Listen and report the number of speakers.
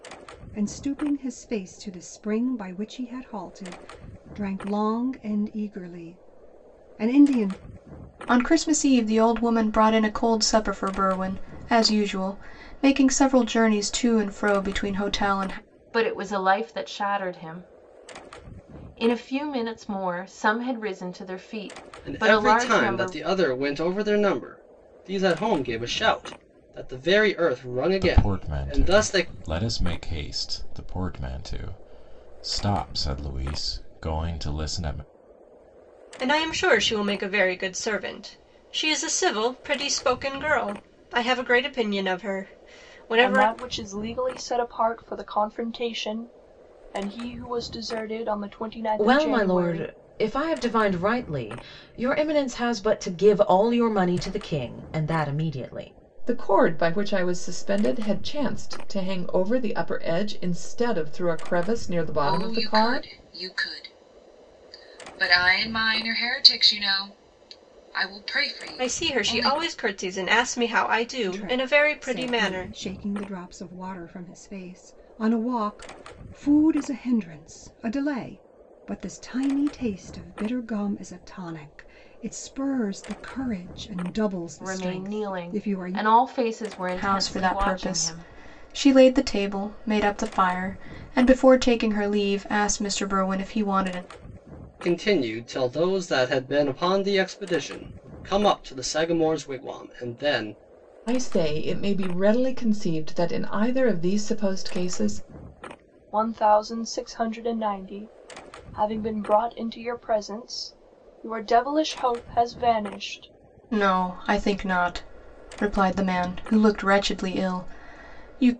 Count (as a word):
ten